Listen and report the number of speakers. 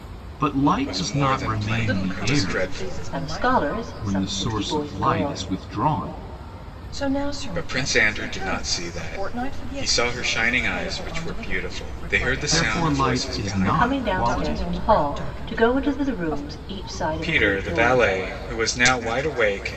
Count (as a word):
four